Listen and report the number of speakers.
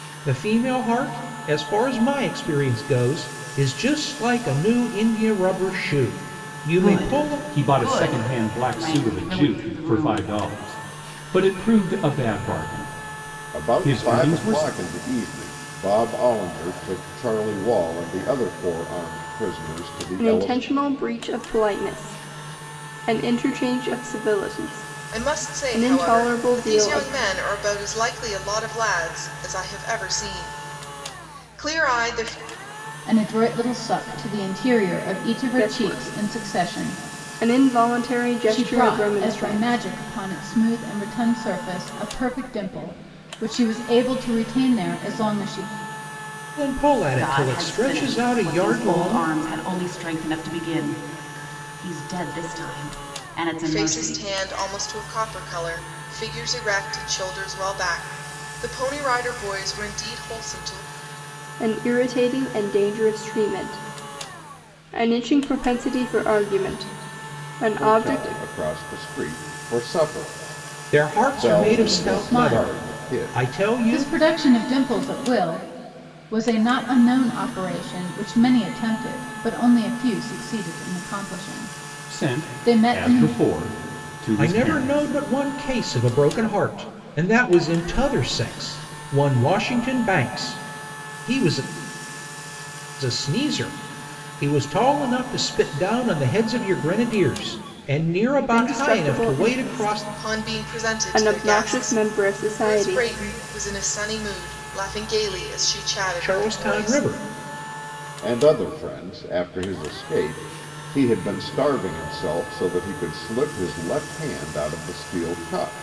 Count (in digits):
7